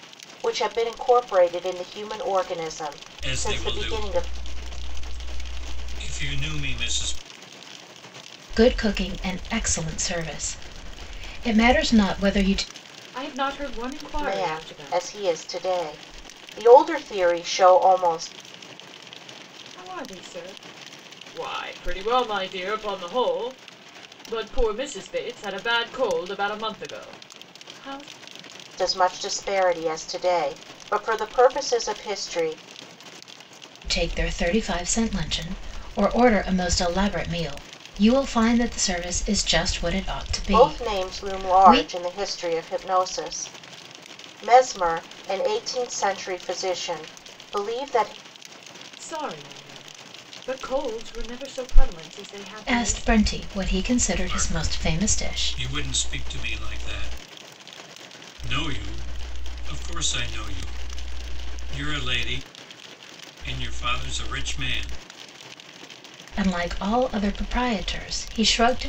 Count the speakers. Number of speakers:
4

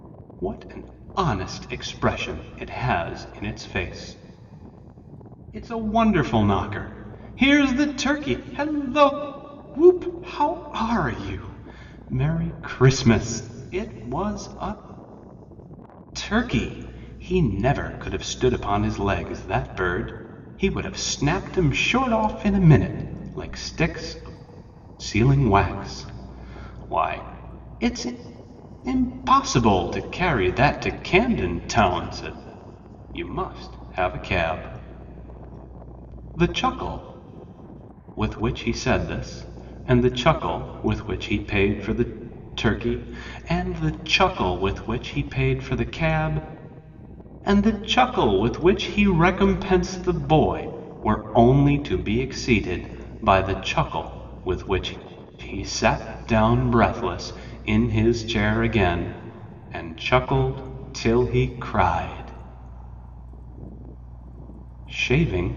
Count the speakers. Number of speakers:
1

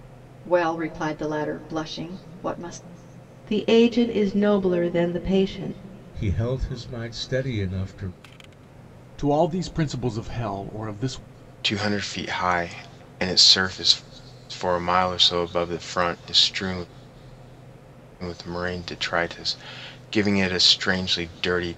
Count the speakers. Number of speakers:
5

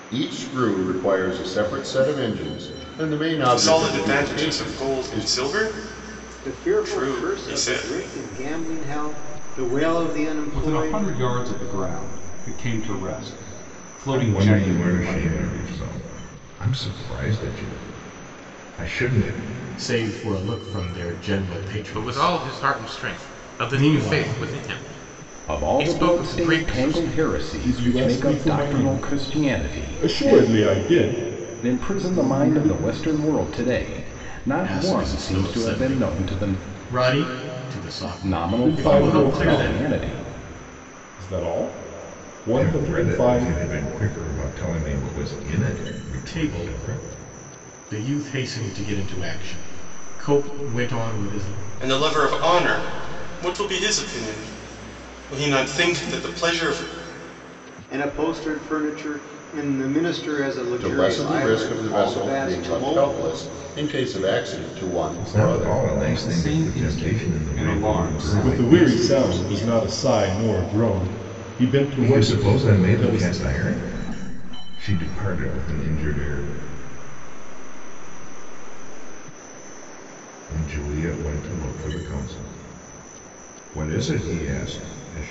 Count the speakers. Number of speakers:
10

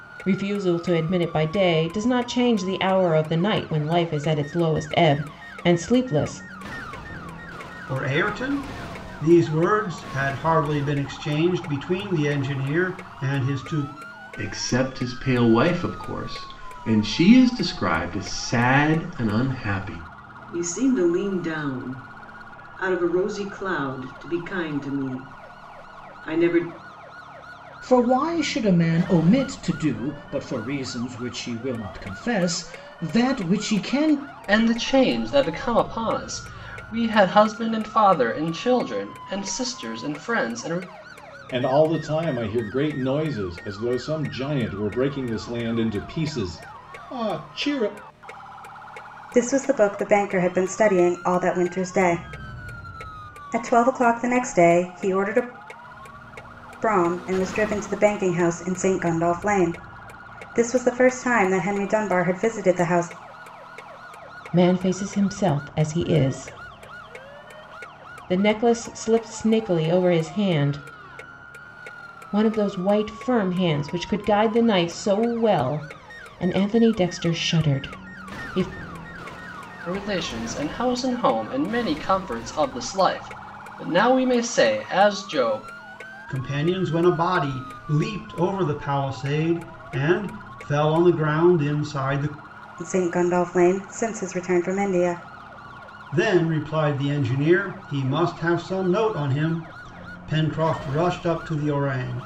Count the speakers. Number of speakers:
8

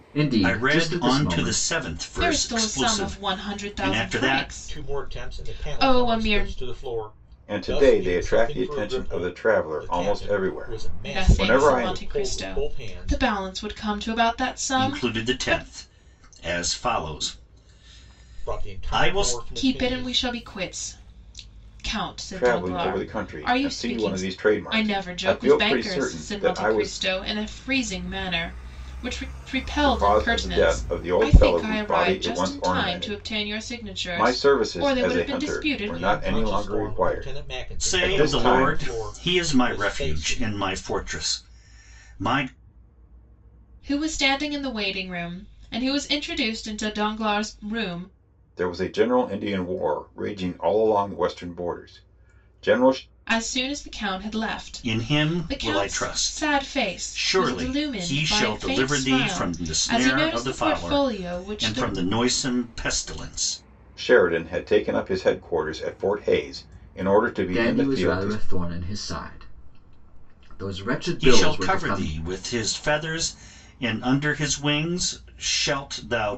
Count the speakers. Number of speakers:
5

